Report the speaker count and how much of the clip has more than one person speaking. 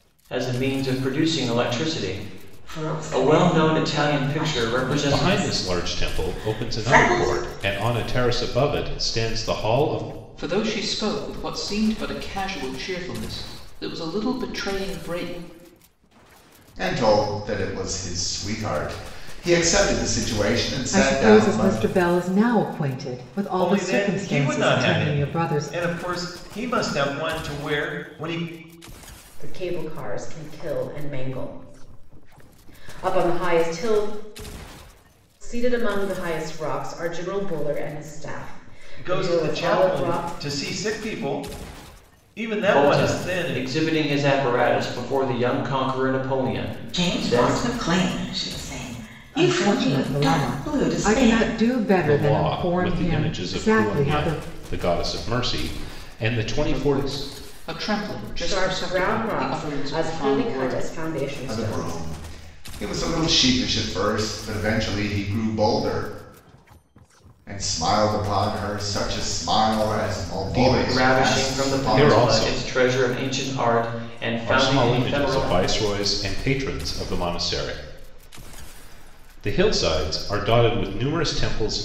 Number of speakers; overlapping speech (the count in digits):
8, about 27%